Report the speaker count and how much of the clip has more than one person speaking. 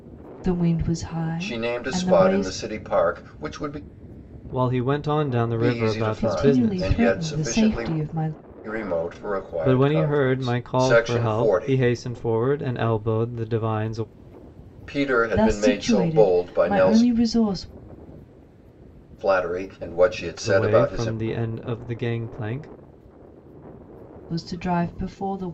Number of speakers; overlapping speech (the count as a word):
three, about 32%